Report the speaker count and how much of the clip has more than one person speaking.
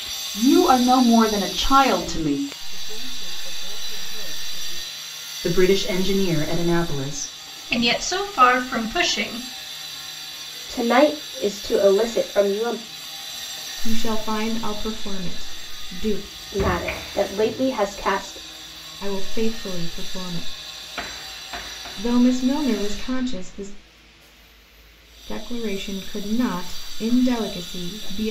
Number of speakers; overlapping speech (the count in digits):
6, no overlap